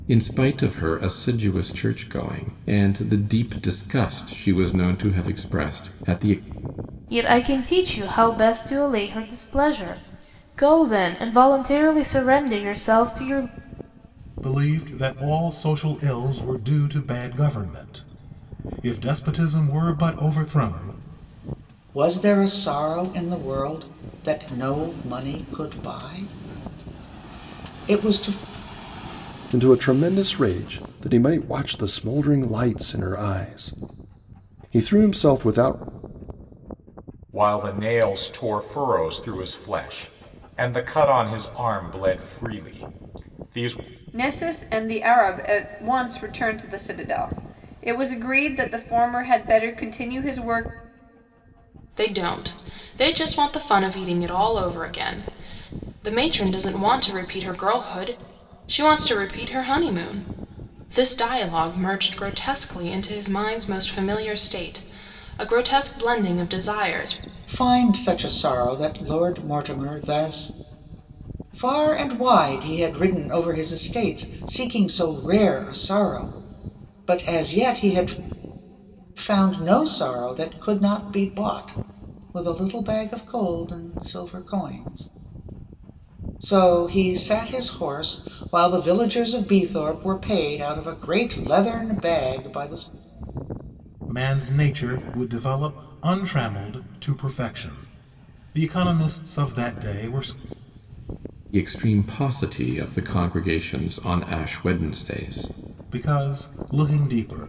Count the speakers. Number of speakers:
8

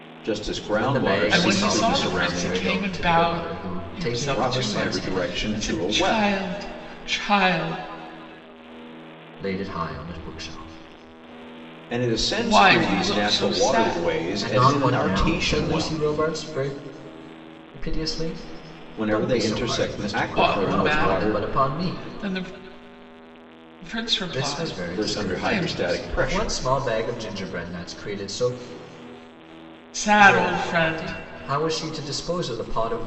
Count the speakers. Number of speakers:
3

